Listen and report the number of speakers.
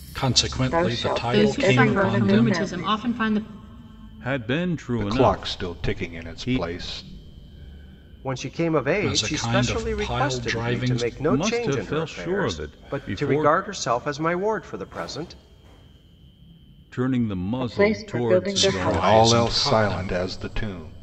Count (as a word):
six